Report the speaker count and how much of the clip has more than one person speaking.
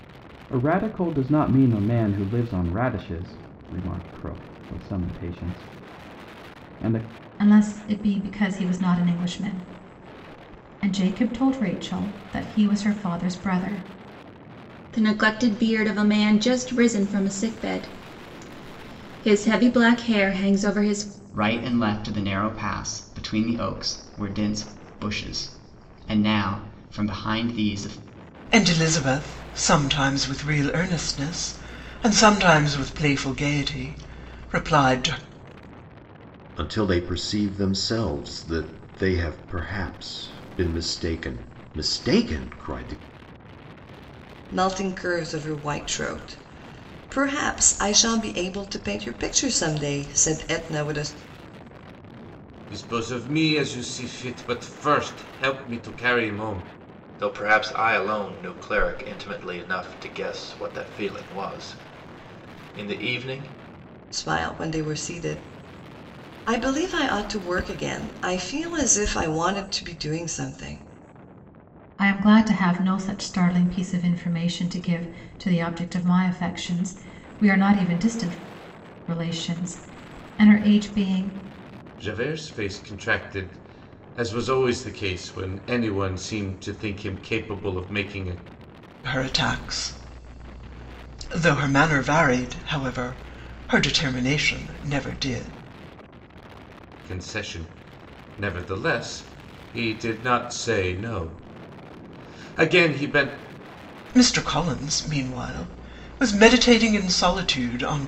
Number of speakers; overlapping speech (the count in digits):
9, no overlap